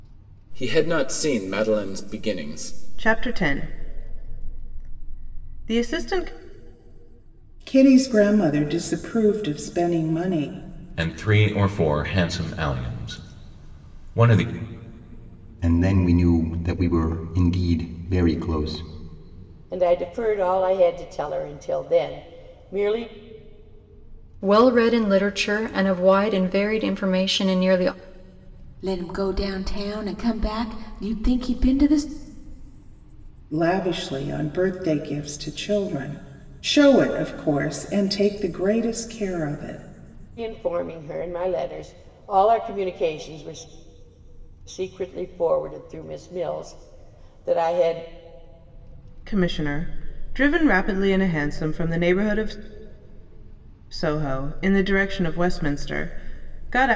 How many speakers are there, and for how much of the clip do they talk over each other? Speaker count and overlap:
8, no overlap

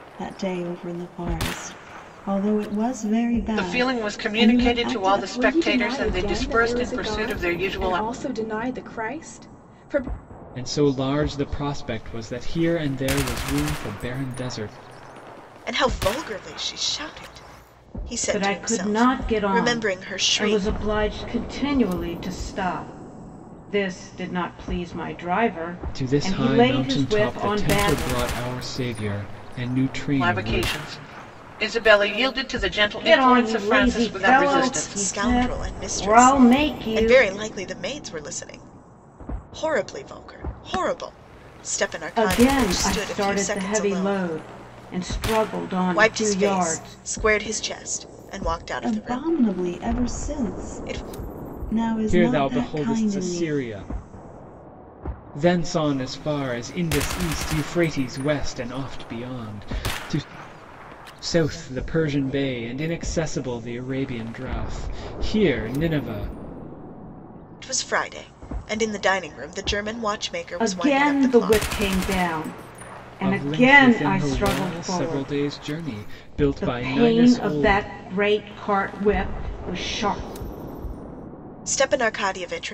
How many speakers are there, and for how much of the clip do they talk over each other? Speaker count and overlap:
6, about 31%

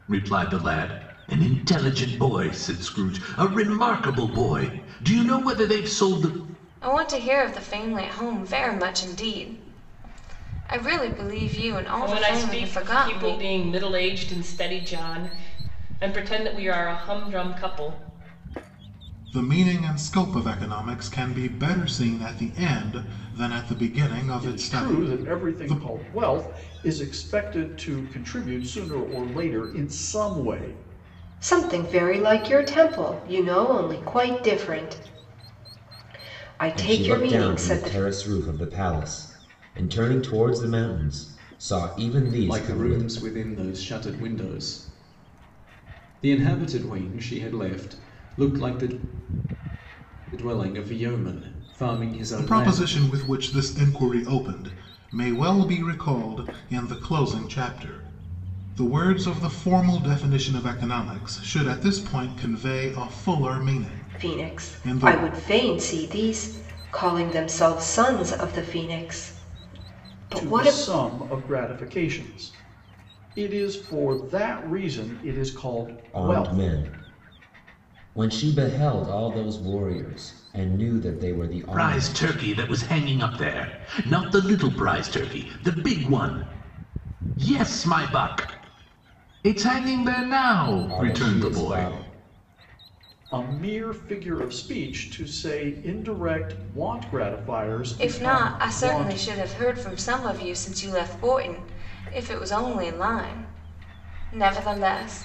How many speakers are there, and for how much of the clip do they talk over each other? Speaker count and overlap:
8, about 10%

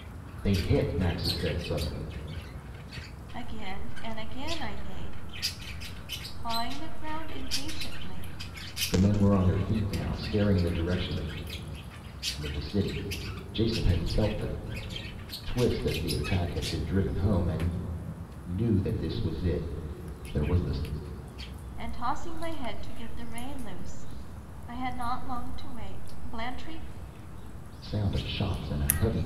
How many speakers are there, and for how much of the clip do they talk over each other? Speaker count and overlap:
2, no overlap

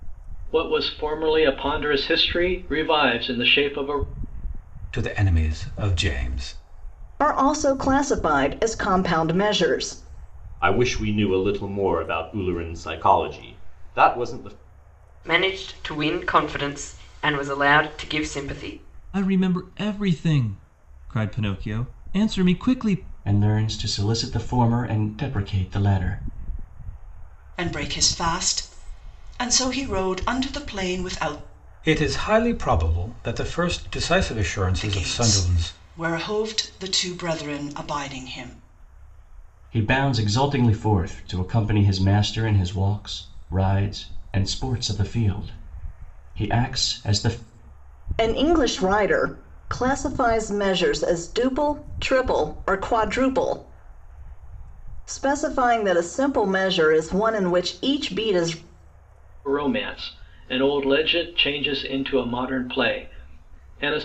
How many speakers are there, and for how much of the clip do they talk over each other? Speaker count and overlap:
8, about 2%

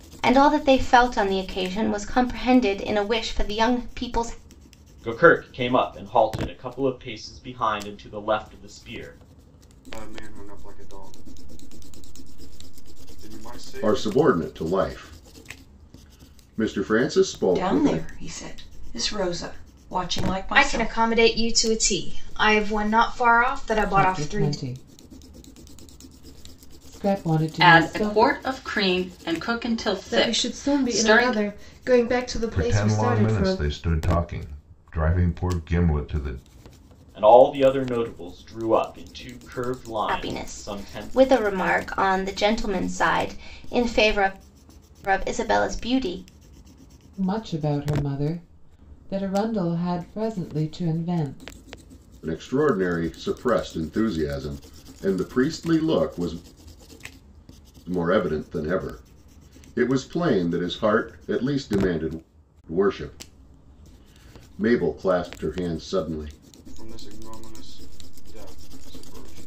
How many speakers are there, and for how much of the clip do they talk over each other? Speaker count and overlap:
10, about 9%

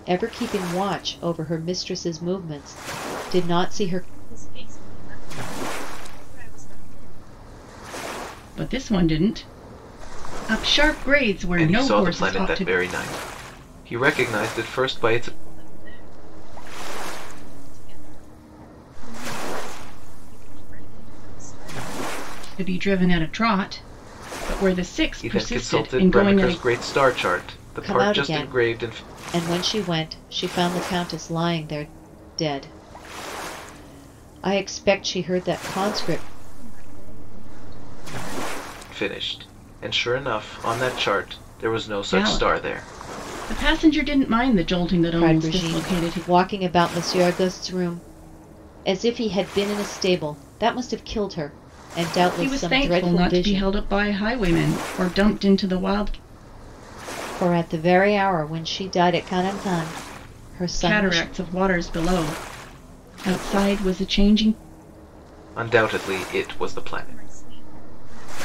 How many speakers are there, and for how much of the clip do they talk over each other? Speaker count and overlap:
4, about 16%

